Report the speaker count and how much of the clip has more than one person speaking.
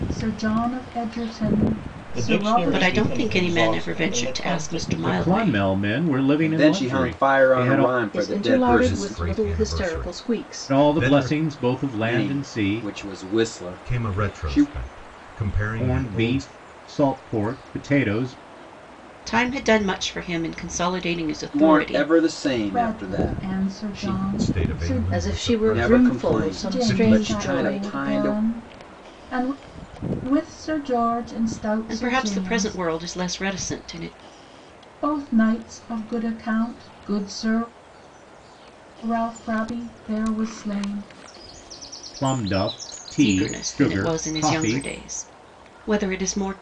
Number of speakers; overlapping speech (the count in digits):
7, about 42%